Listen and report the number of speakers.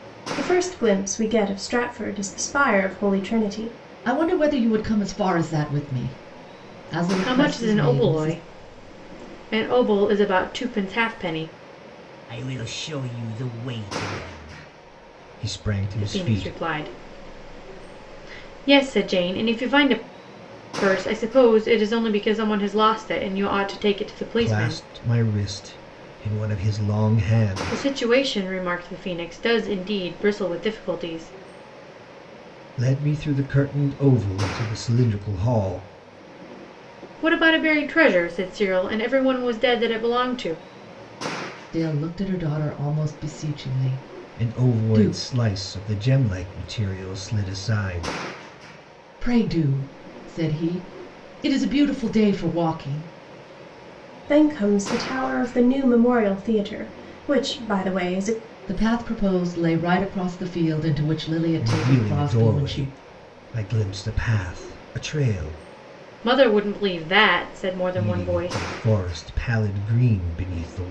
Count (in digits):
4